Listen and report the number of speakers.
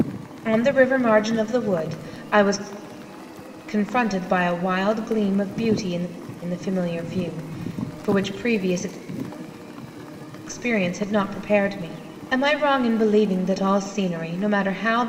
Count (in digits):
1